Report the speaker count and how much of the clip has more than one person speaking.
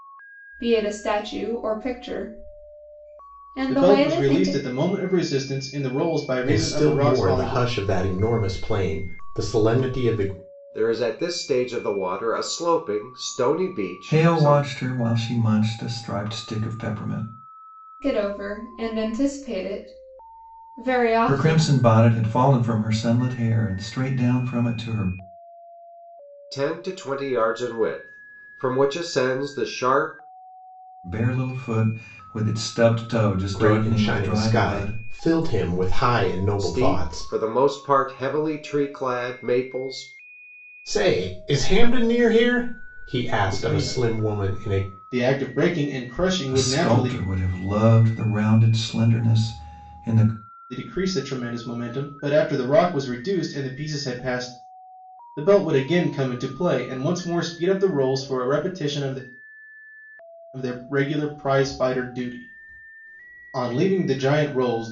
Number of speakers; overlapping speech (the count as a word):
five, about 12%